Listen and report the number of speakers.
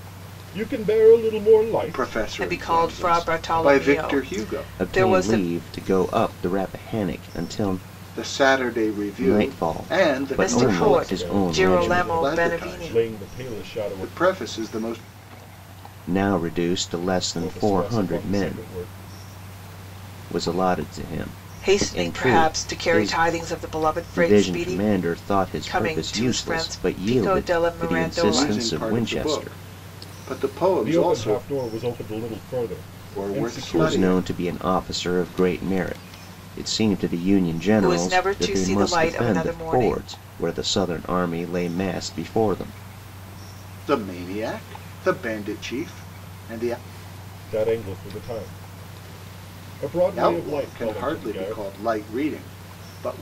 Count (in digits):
4